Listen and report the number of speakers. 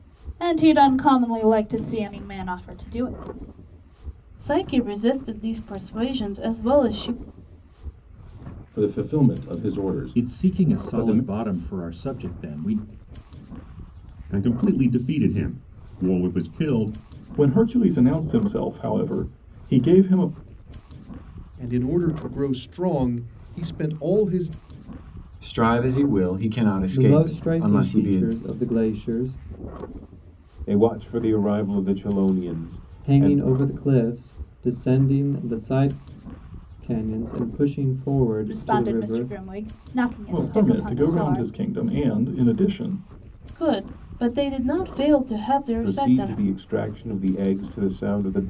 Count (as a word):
ten